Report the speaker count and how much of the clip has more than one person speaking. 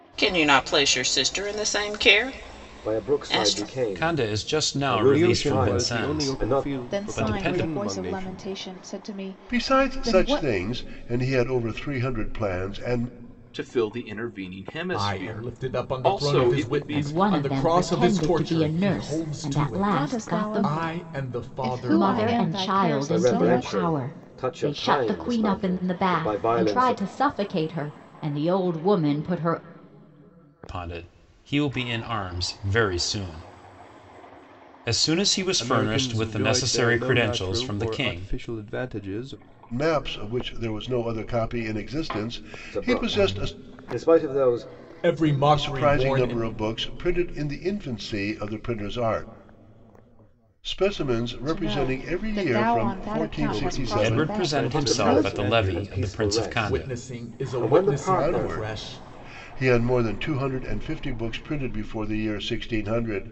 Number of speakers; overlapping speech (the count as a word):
nine, about 51%